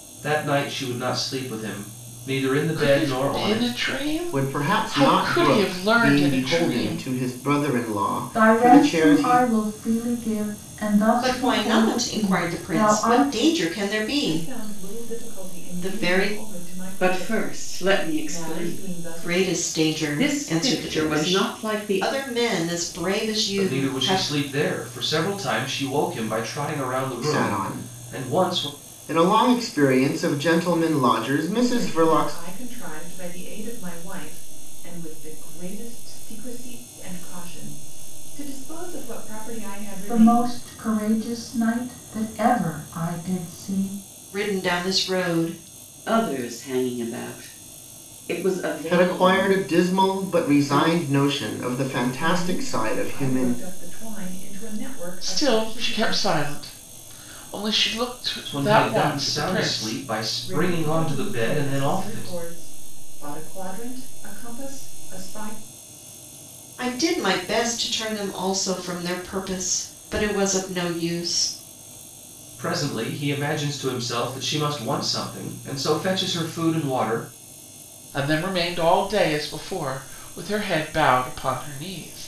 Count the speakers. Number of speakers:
7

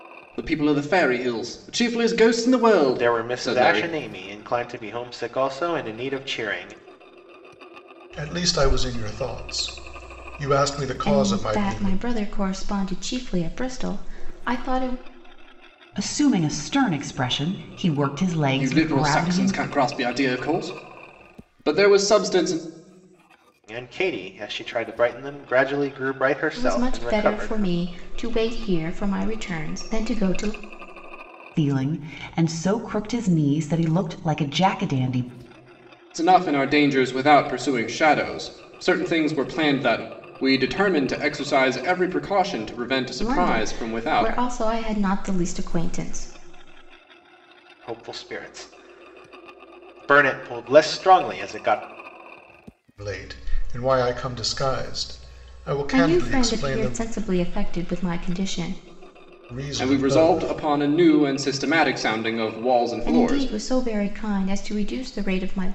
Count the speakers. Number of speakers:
5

